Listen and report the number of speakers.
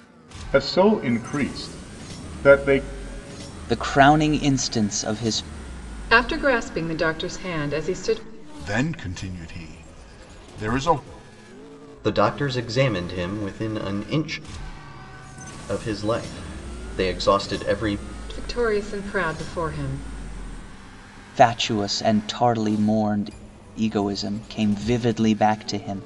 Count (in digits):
5